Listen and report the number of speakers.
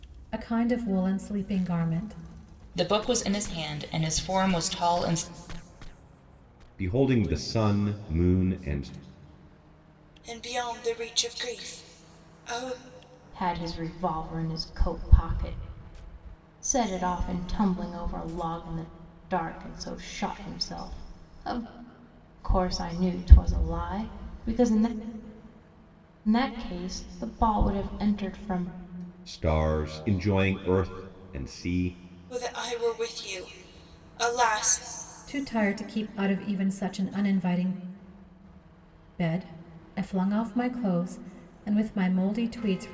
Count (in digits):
5